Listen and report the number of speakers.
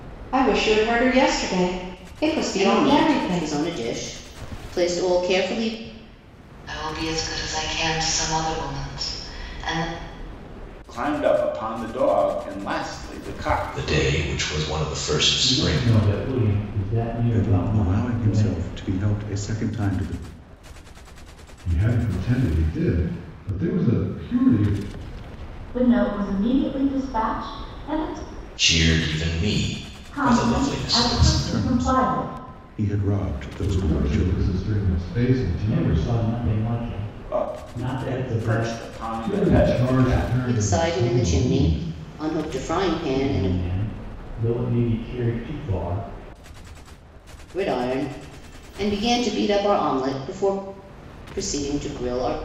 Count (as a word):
nine